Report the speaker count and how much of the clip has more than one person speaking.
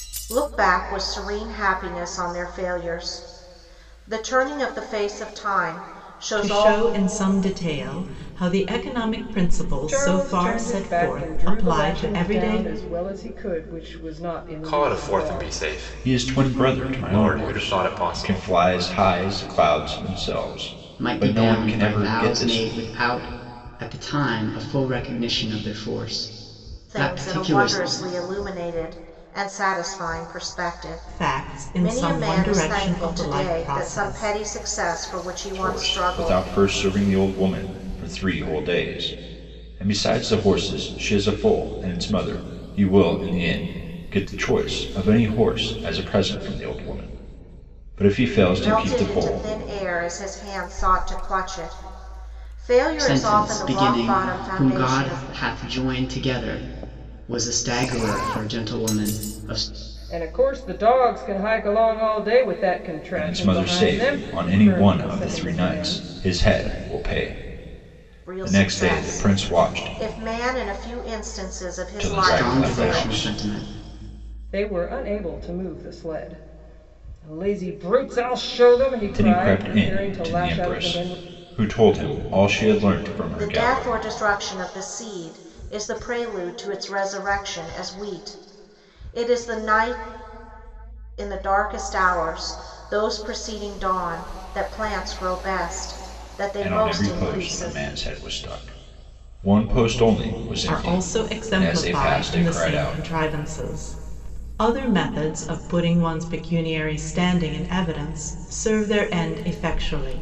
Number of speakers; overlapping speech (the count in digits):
6, about 27%